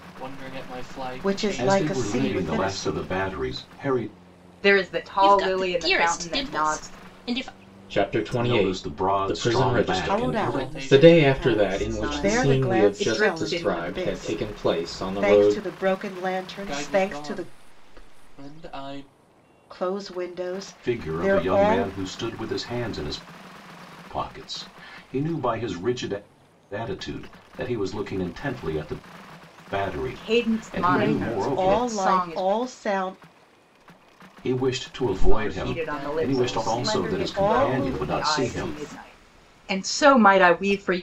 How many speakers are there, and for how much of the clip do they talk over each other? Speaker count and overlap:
six, about 46%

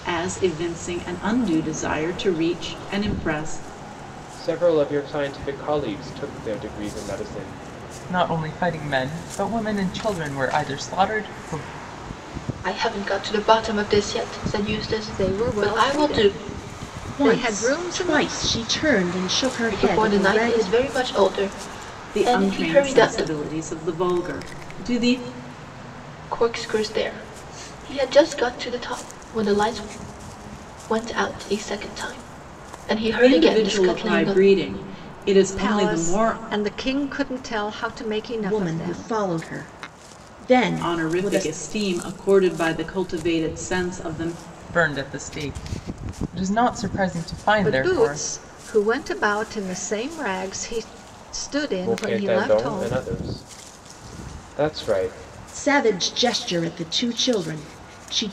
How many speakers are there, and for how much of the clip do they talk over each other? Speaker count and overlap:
six, about 17%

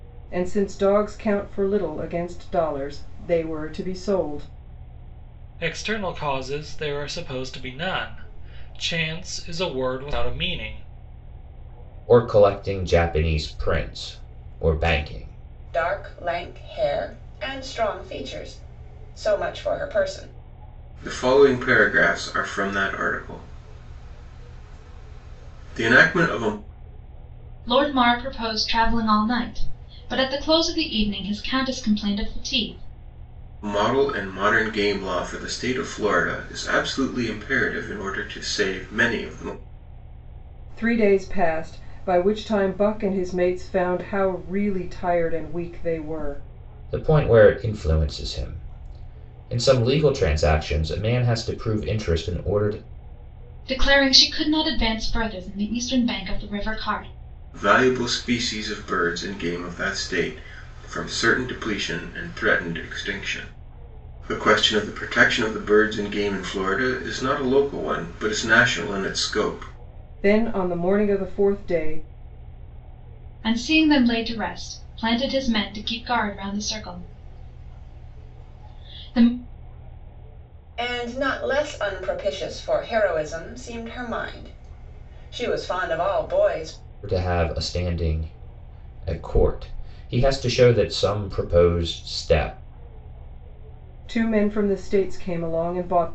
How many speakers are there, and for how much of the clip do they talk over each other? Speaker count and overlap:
six, no overlap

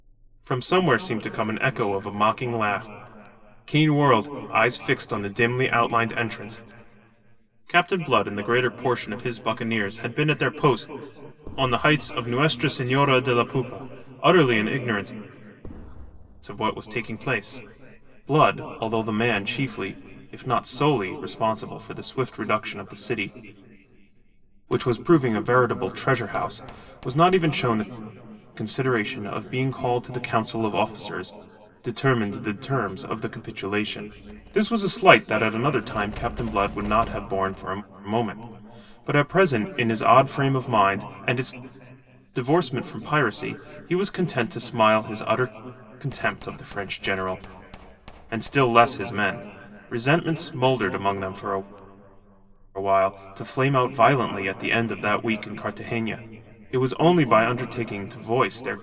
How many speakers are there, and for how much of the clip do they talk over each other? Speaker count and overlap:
one, no overlap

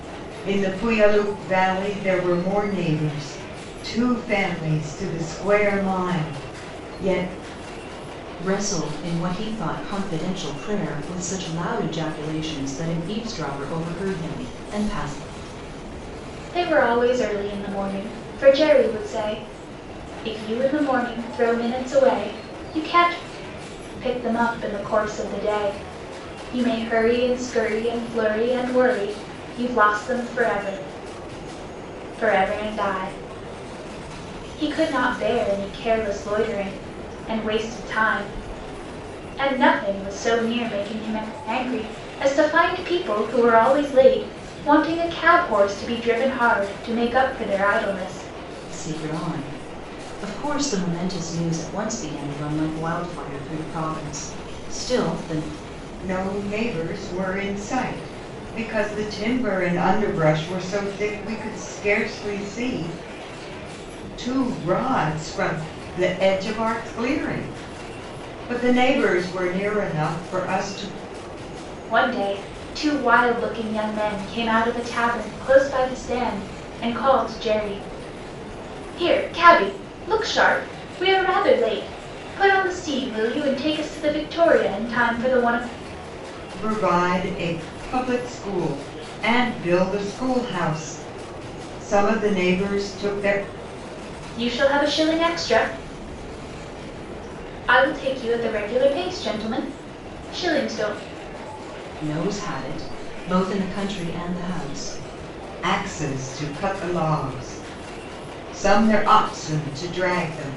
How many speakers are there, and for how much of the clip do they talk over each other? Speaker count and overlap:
three, no overlap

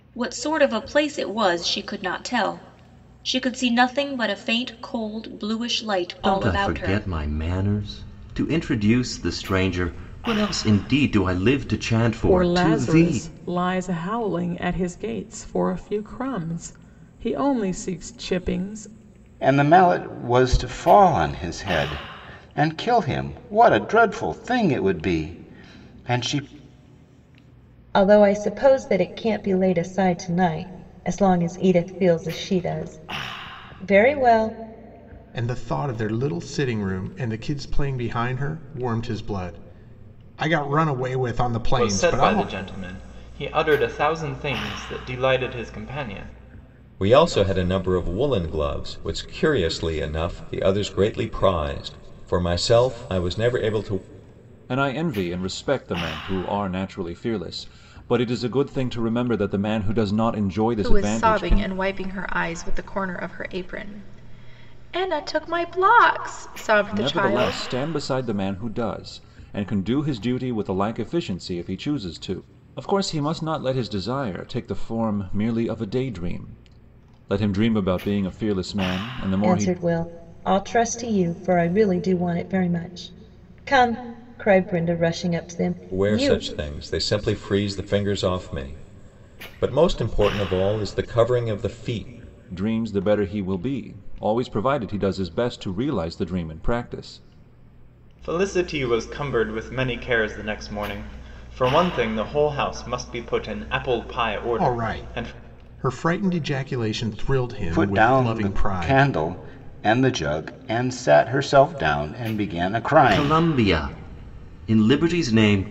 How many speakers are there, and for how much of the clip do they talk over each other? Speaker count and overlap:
ten, about 7%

